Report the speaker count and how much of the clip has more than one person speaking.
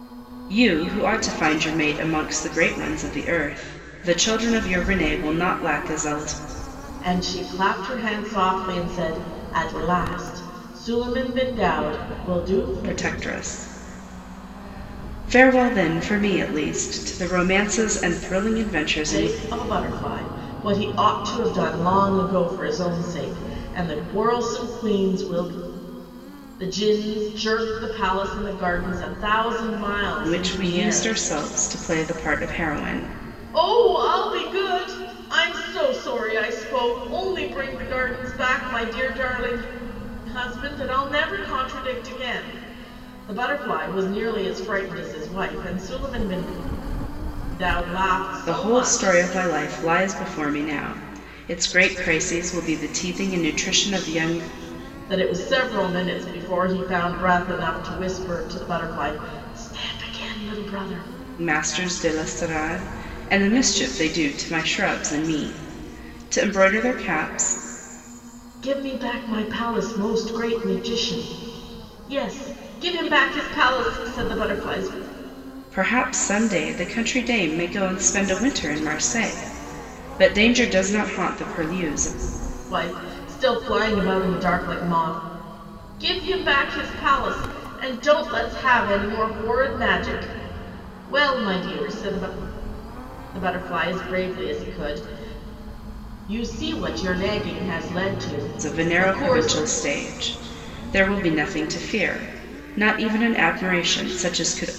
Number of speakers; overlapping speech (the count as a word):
two, about 3%